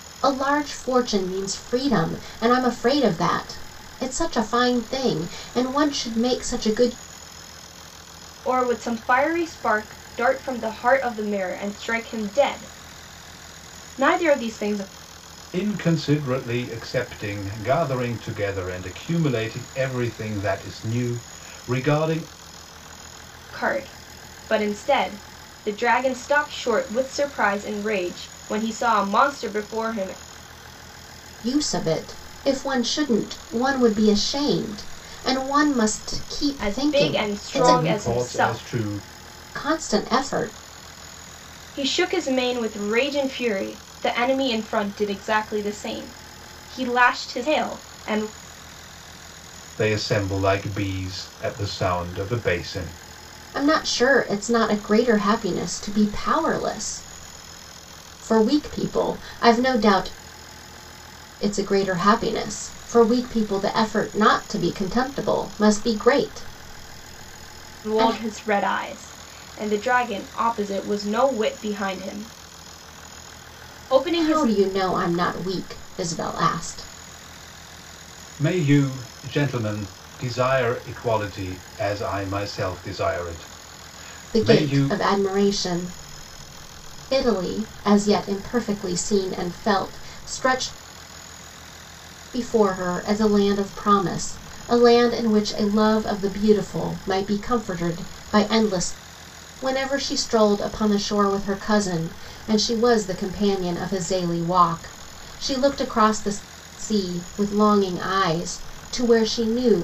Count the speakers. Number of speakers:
3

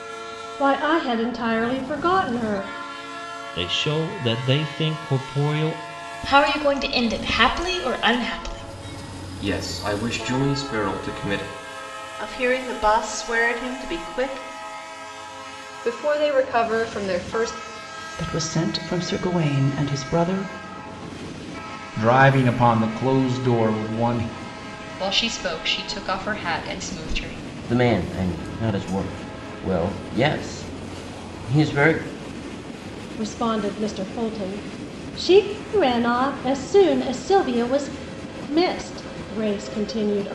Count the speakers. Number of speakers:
10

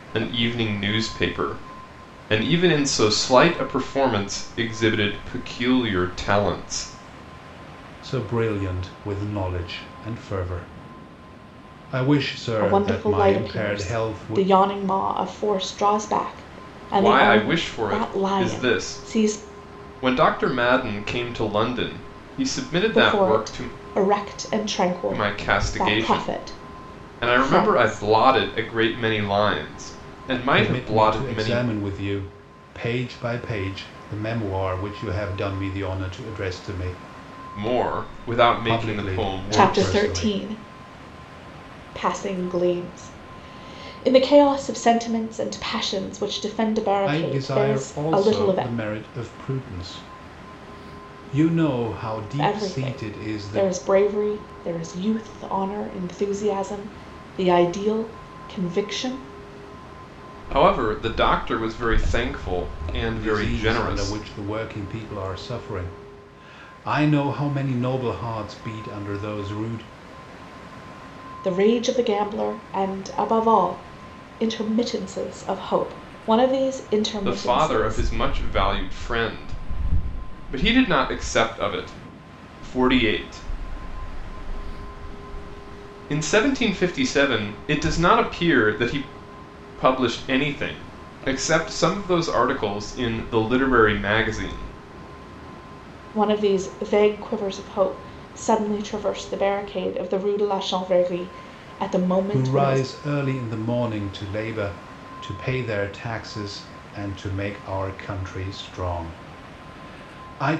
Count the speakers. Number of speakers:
3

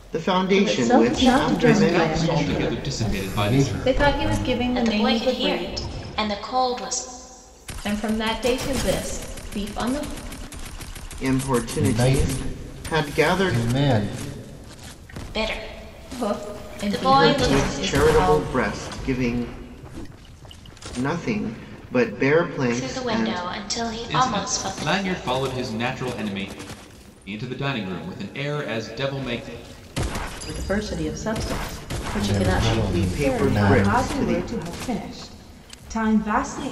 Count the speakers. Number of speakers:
7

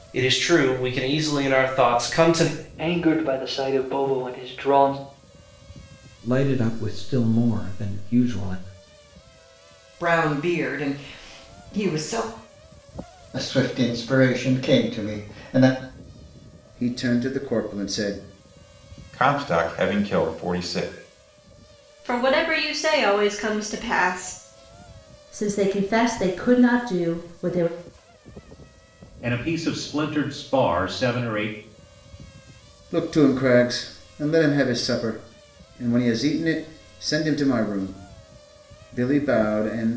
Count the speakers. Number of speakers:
10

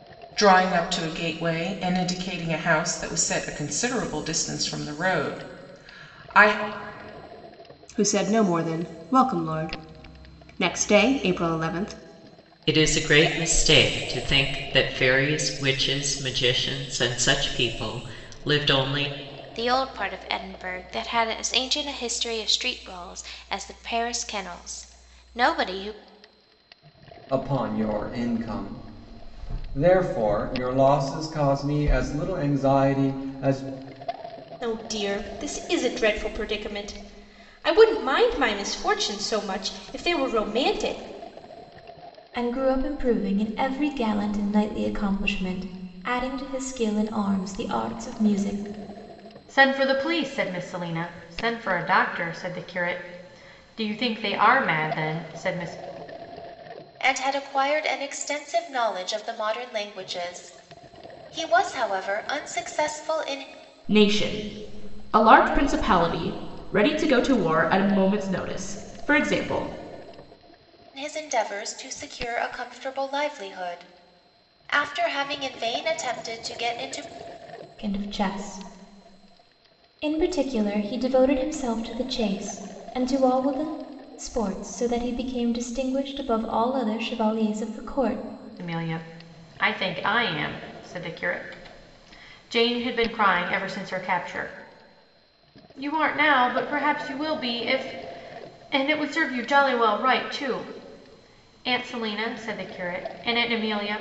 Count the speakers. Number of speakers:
10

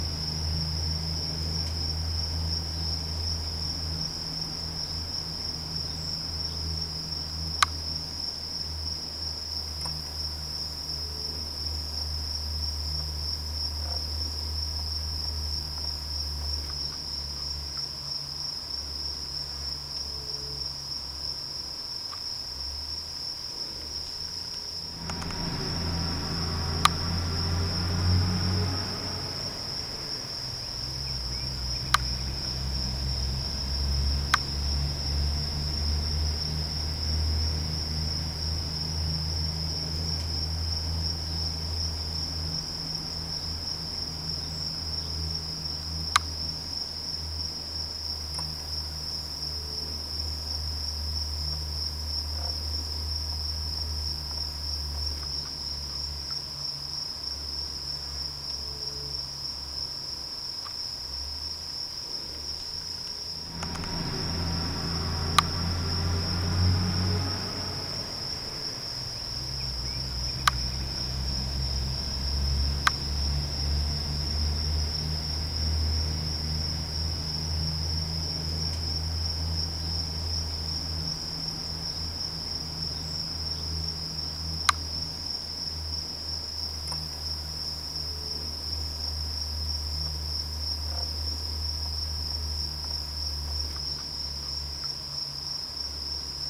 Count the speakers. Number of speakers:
0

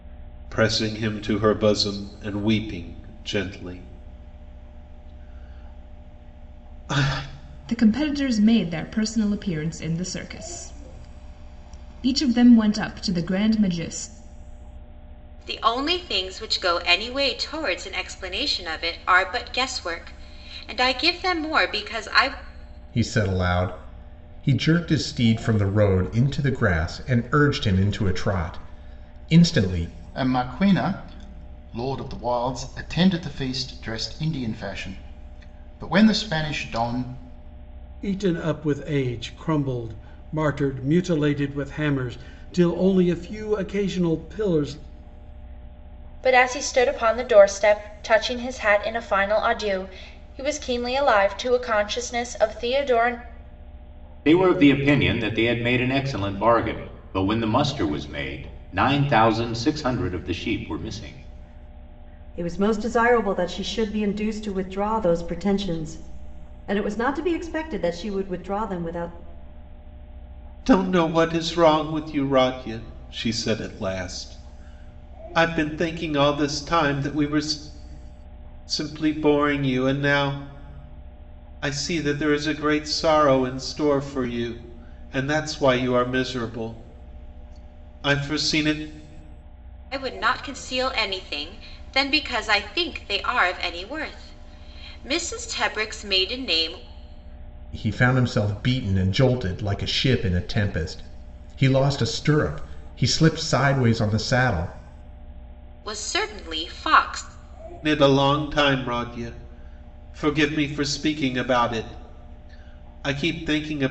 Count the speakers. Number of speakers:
9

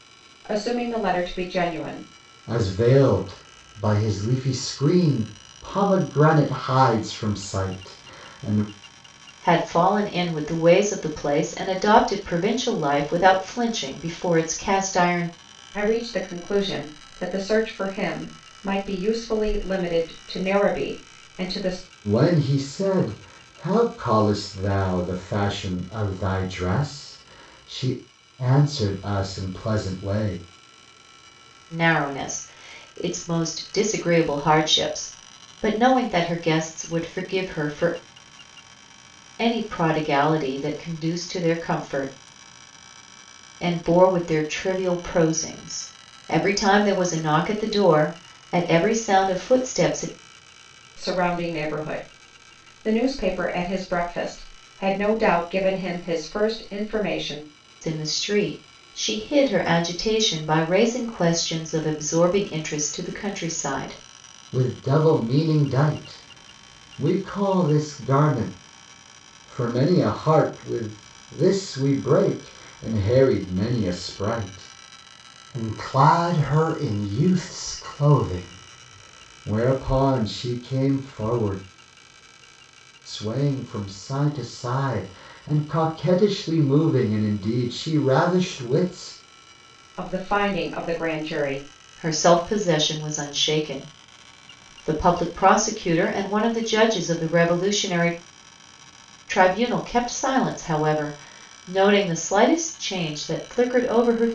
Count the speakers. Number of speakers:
3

